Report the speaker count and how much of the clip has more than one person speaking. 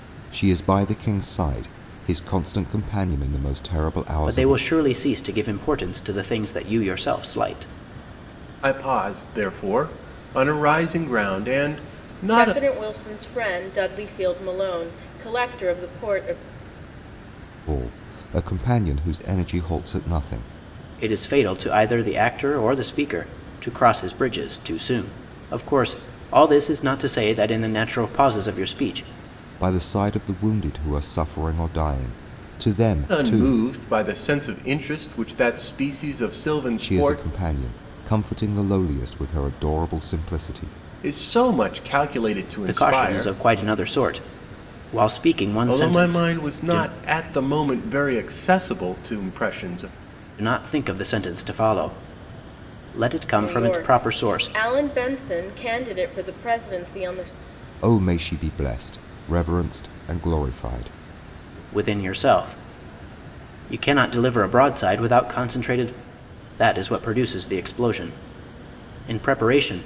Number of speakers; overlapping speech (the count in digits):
4, about 7%